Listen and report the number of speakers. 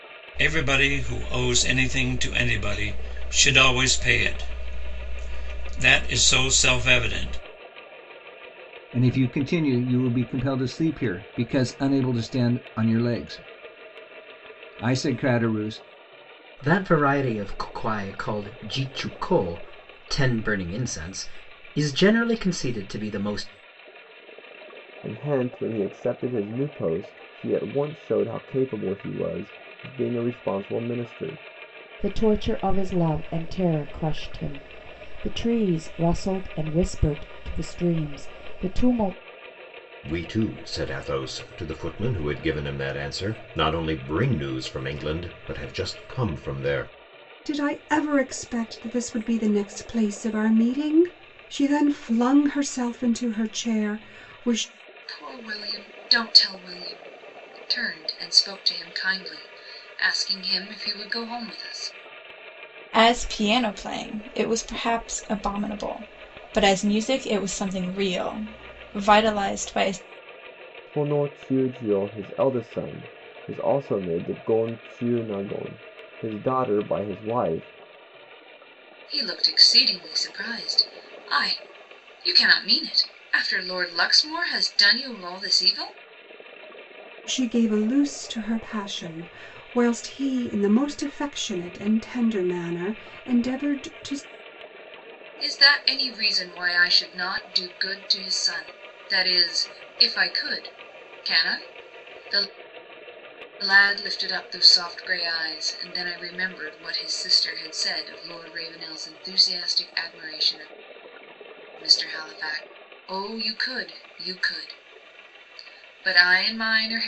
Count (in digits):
9